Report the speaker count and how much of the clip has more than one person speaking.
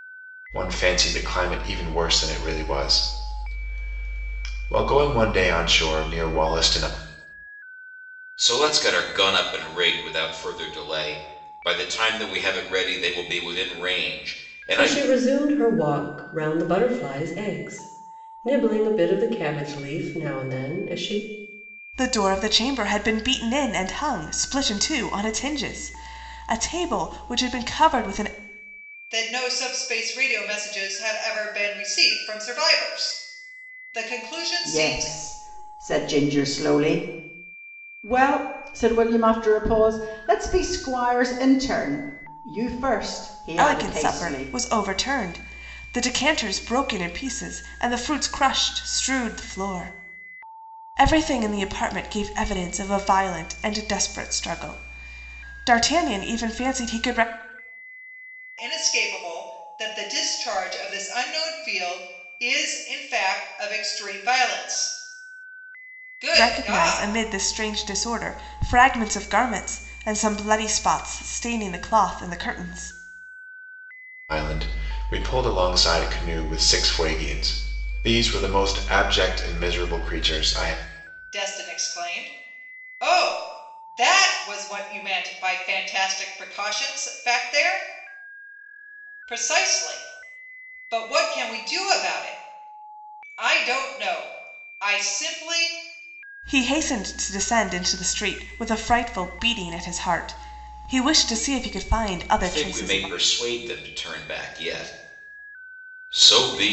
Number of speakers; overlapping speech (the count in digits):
6, about 3%